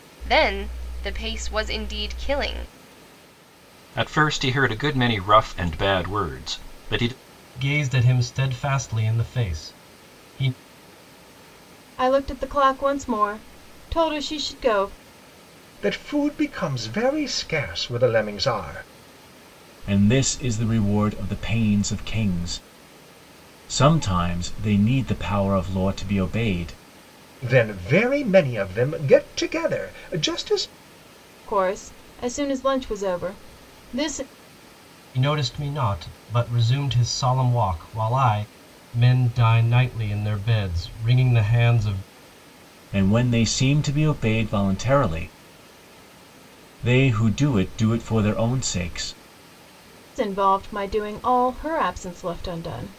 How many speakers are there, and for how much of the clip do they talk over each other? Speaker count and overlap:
six, no overlap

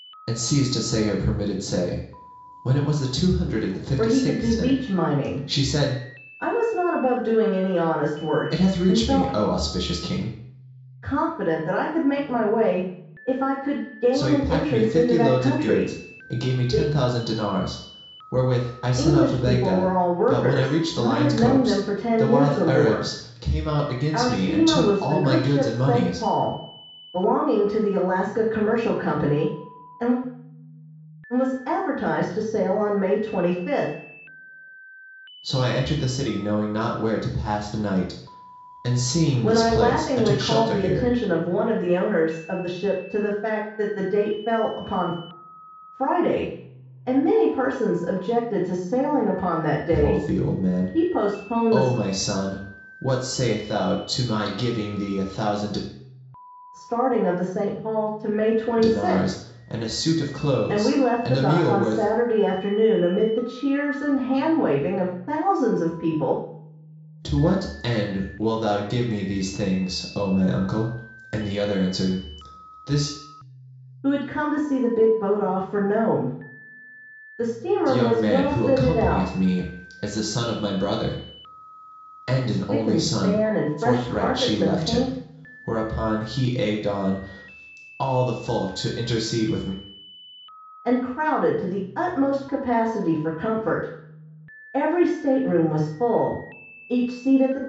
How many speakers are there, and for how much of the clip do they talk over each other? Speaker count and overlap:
two, about 22%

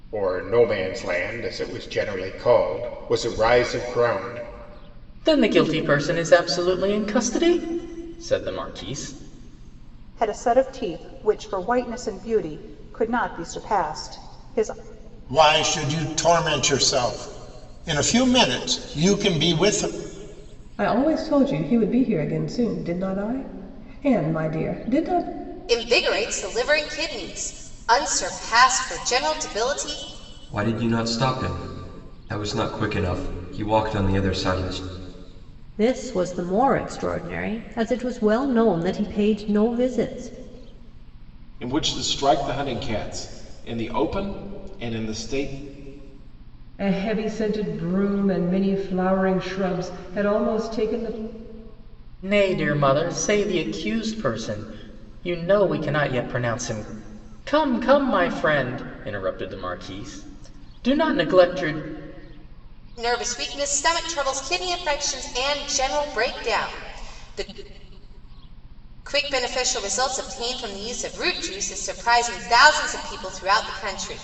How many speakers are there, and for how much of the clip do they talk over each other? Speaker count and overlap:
ten, no overlap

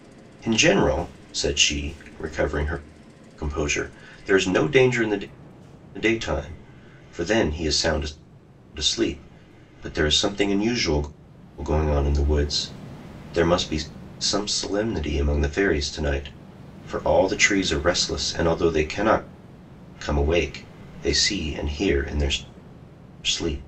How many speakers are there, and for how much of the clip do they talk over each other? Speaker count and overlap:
one, no overlap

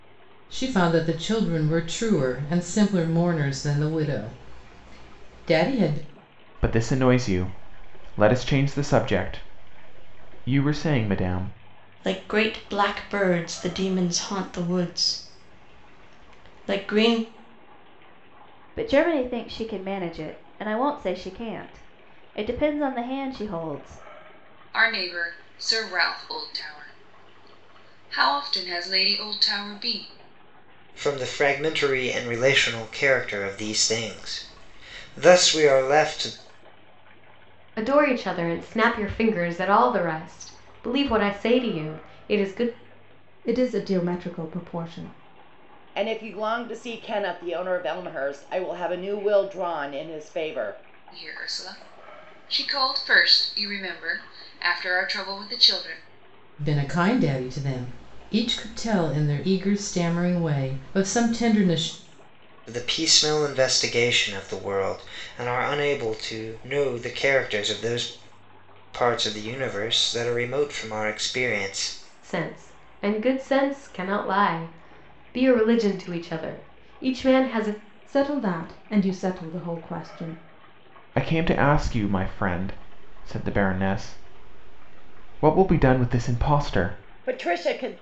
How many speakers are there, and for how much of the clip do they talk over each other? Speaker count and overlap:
nine, no overlap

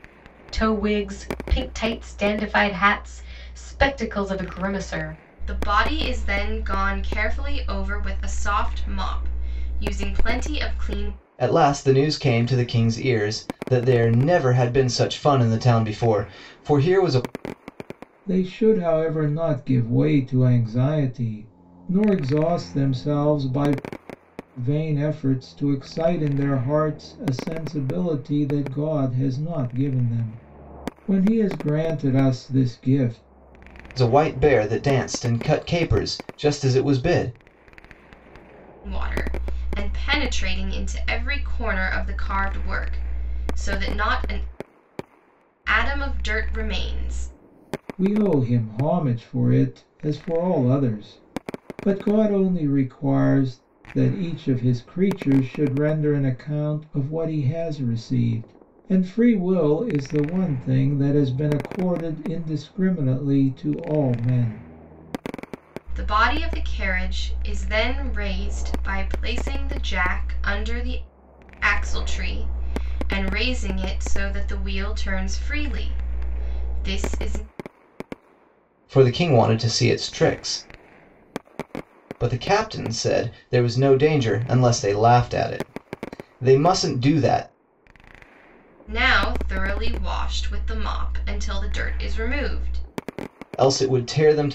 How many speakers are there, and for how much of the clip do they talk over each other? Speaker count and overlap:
four, no overlap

